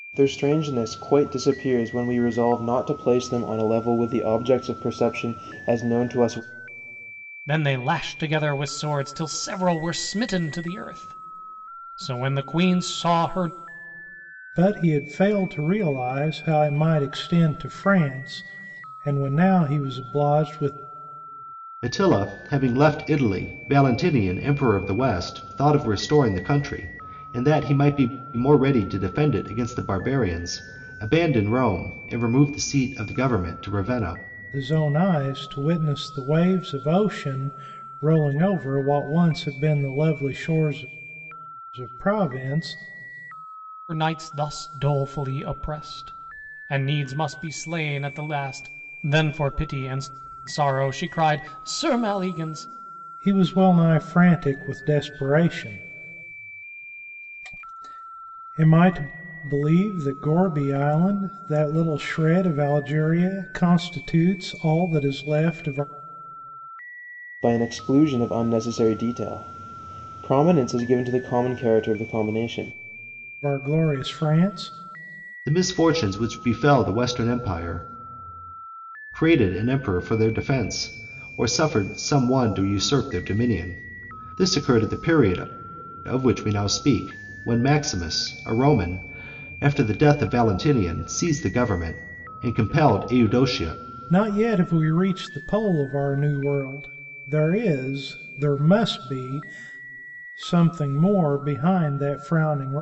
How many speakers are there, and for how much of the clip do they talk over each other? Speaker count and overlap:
four, no overlap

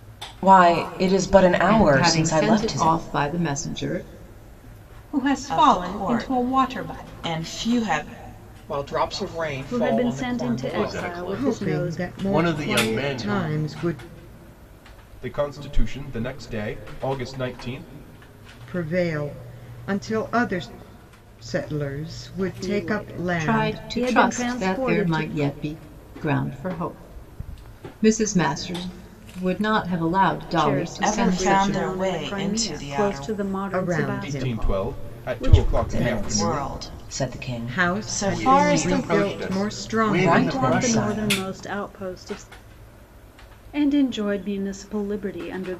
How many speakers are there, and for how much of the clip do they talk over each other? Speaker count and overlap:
nine, about 44%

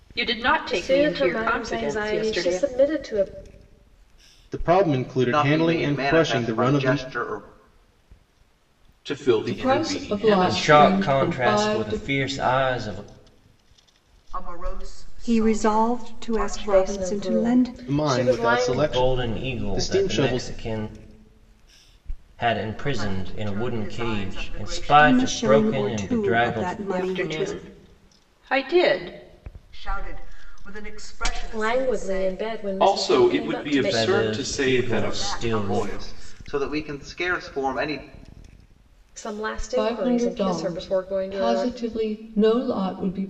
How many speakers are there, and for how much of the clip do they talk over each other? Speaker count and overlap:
nine, about 53%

